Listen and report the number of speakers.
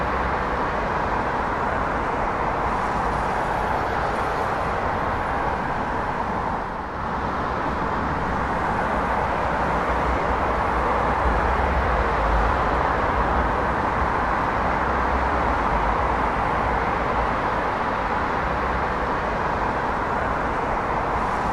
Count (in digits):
0